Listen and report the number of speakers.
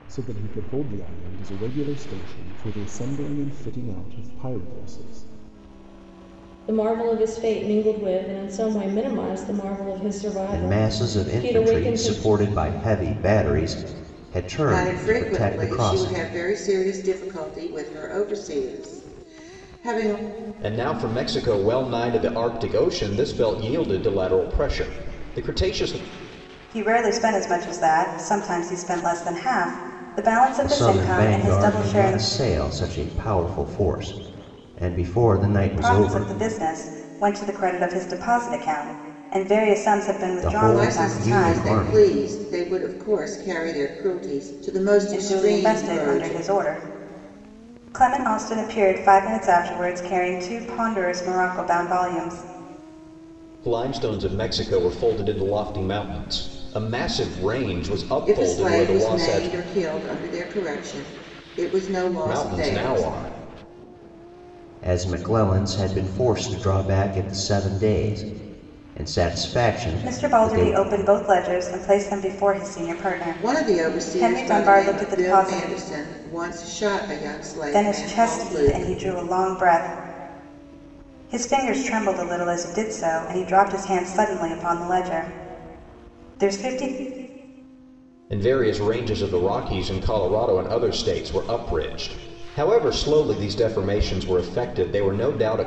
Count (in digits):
6